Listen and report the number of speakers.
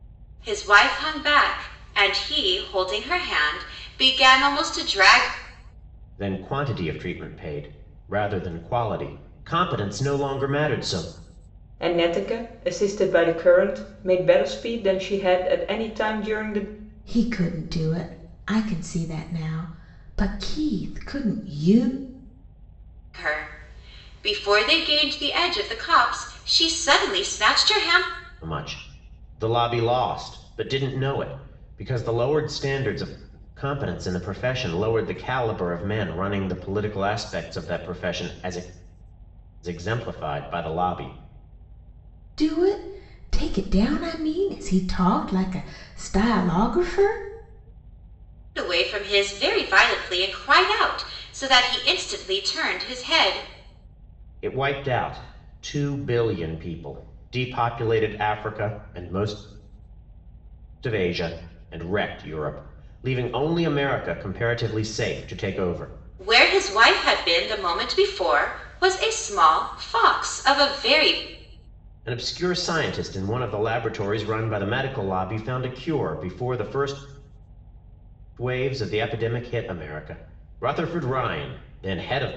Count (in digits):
4